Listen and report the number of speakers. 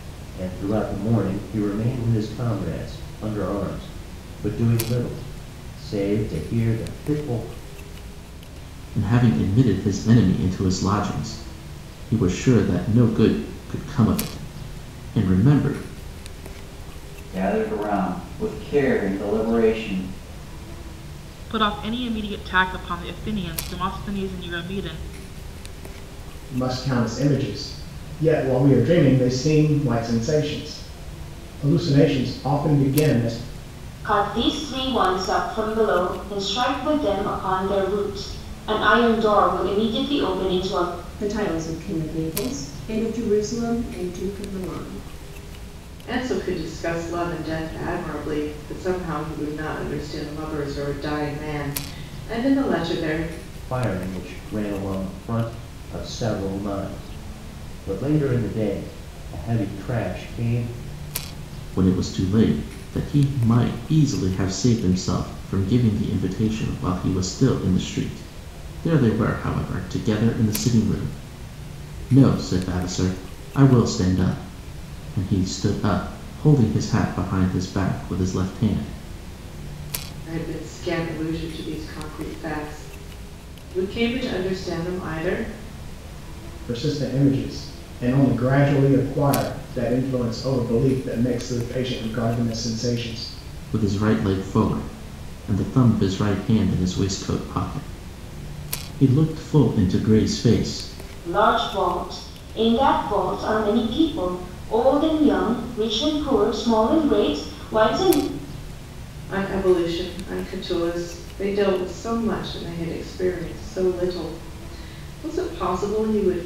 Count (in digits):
8